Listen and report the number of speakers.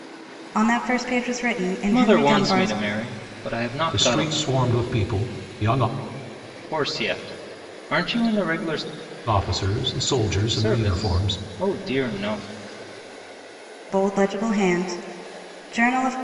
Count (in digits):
3